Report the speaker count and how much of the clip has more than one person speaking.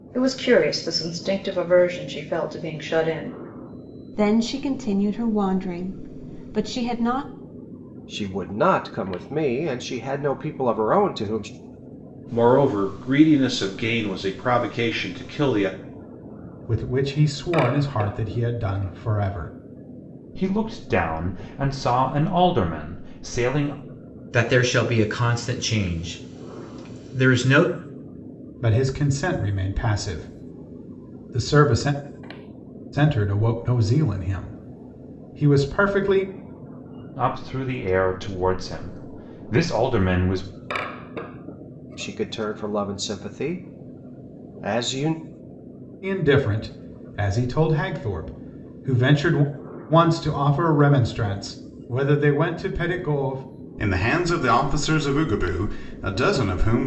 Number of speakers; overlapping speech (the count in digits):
7, no overlap